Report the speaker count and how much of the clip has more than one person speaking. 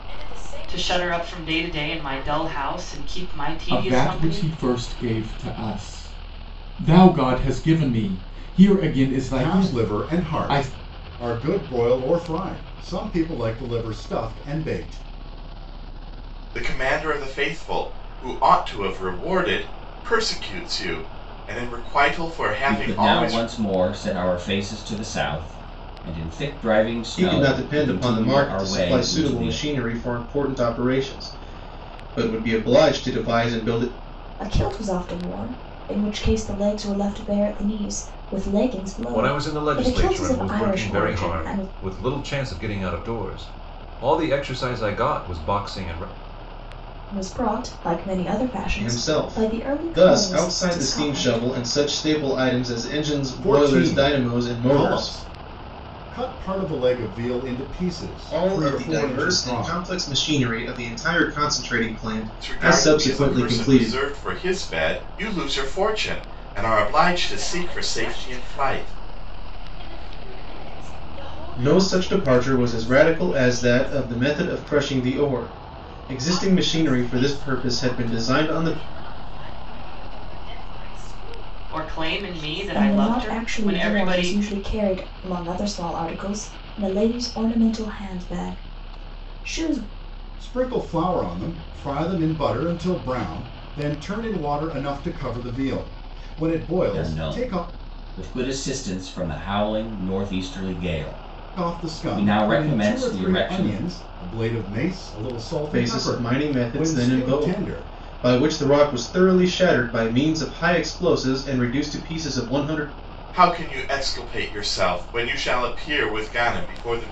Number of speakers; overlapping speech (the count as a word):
nine, about 28%